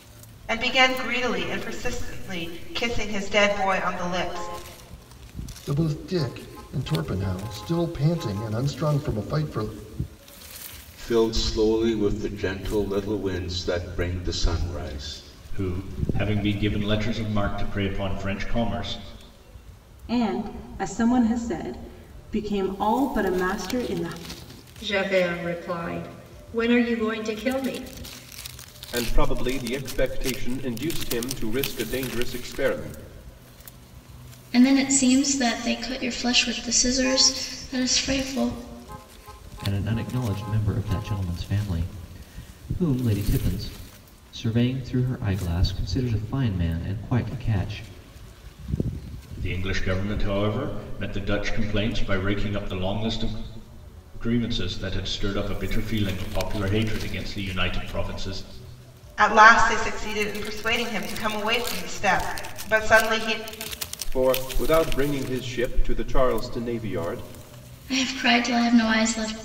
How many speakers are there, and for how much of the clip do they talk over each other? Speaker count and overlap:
nine, no overlap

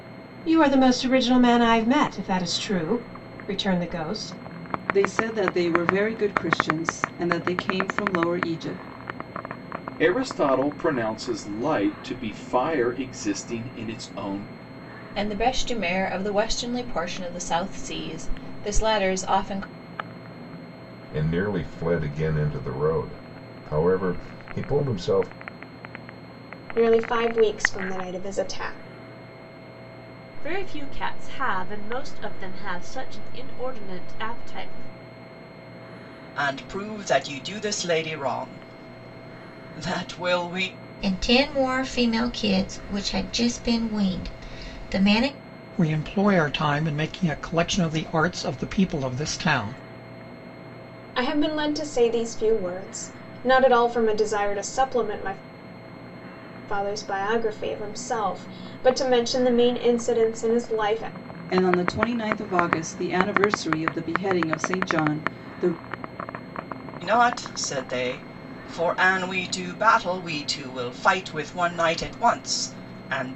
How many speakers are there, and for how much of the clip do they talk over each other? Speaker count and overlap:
ten, no overlap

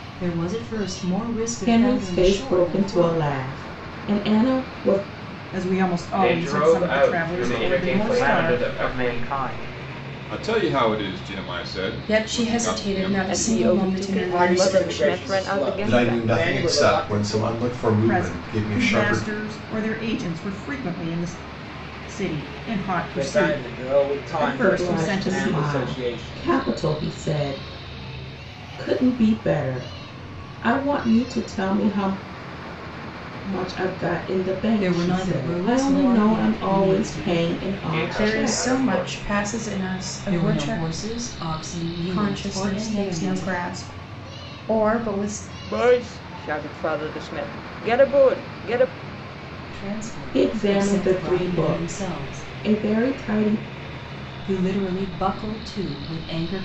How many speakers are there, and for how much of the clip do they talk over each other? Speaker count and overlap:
ten, about 42%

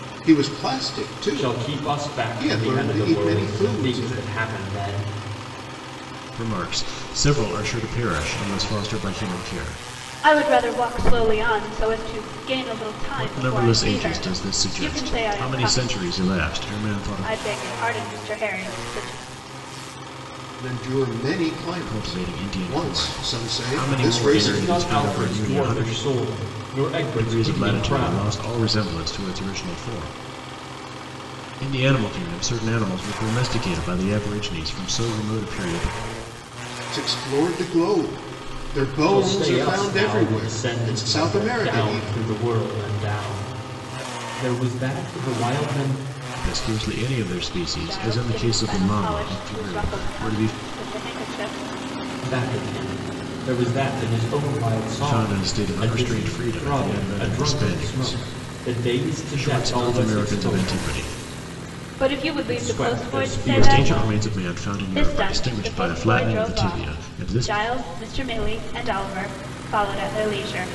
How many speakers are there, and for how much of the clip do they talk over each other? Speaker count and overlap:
four, about 38%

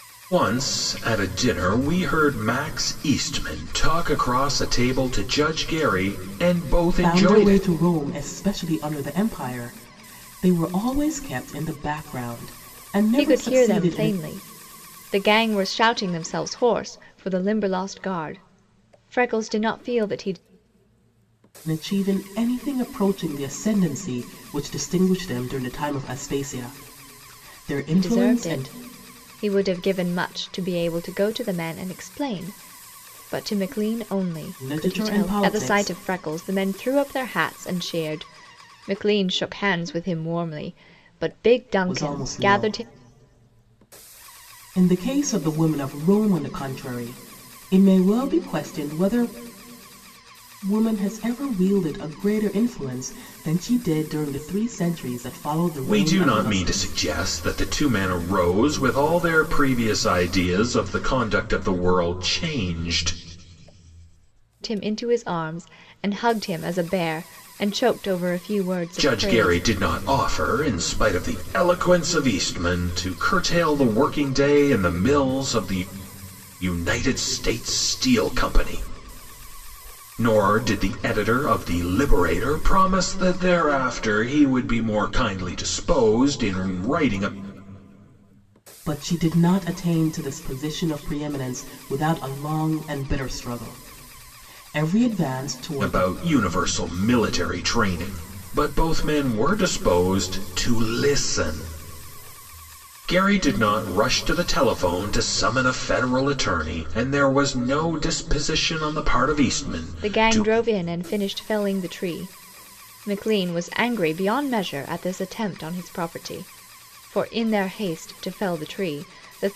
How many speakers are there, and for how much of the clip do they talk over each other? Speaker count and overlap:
three, about 6%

